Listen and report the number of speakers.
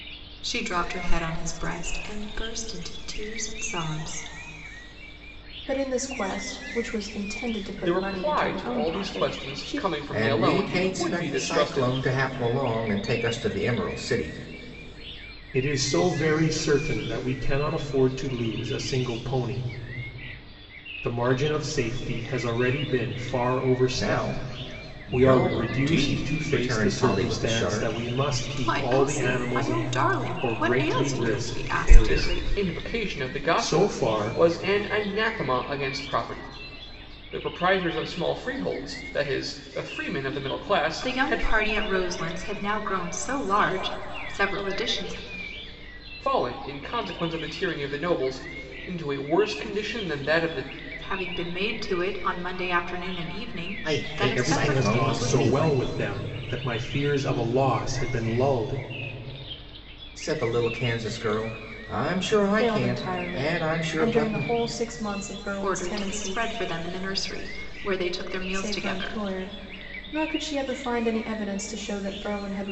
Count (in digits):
5